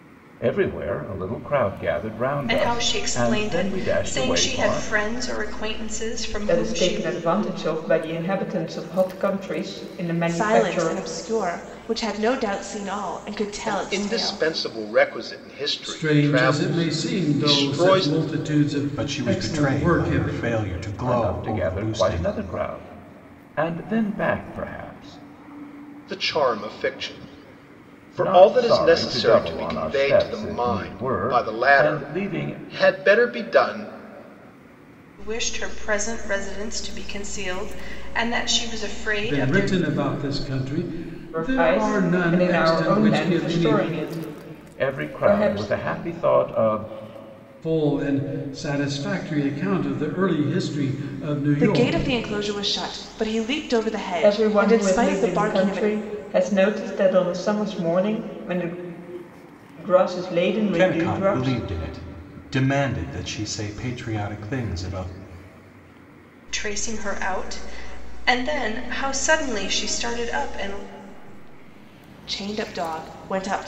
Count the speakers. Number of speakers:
seven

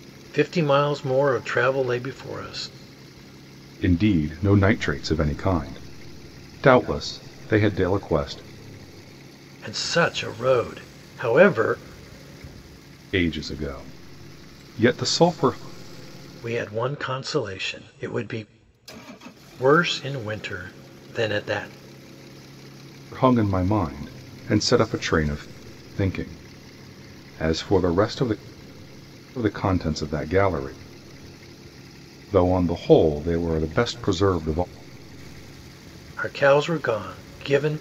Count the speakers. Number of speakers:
two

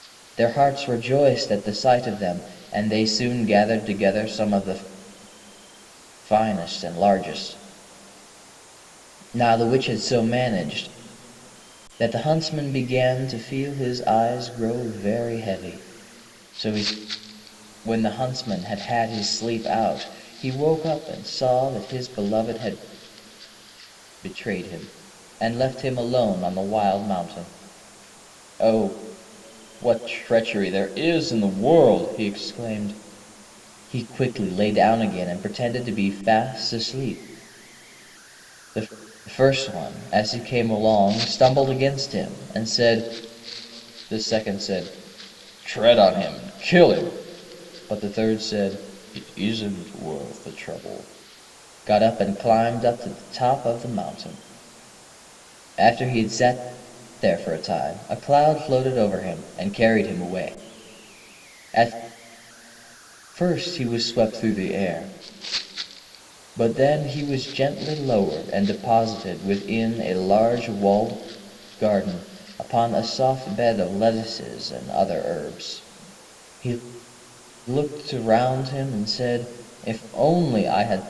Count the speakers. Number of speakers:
one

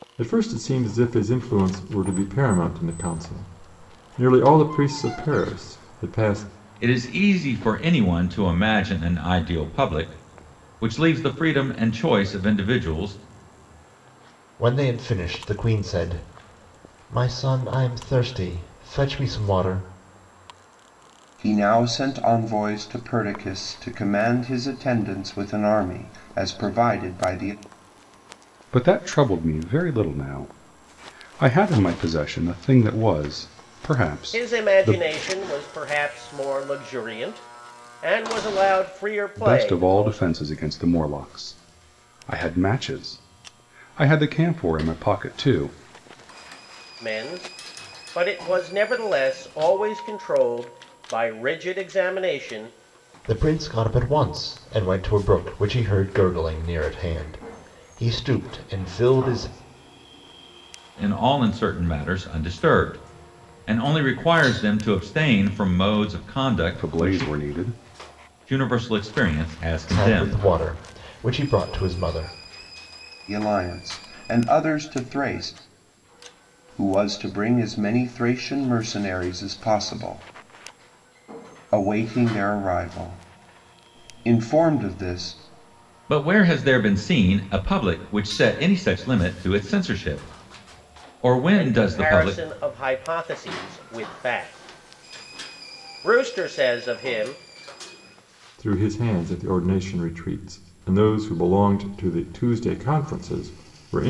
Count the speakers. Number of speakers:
six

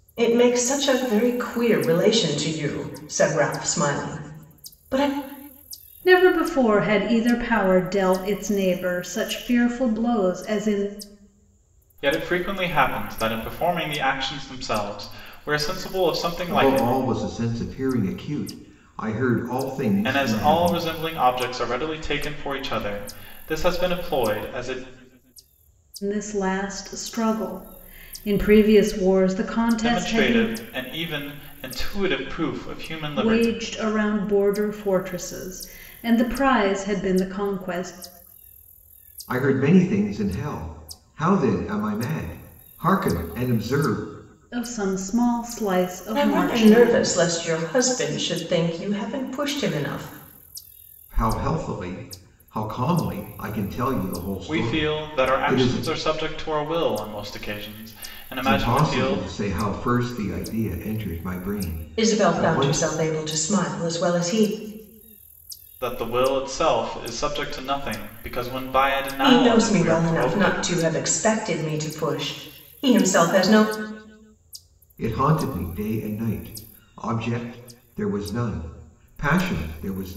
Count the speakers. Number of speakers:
four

